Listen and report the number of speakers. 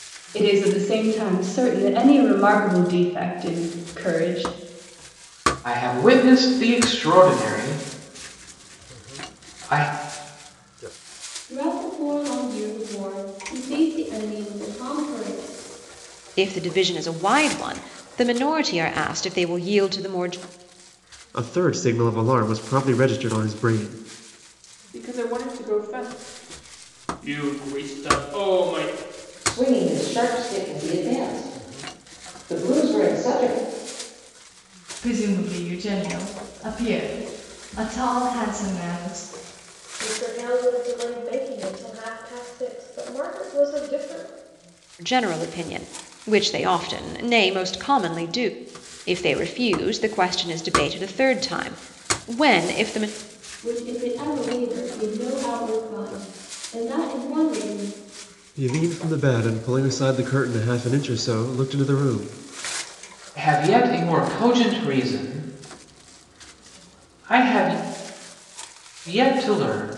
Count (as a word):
nine